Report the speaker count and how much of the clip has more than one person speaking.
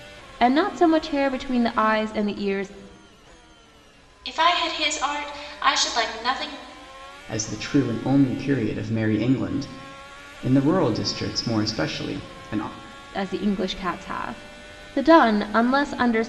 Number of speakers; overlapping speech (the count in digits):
3, no overlap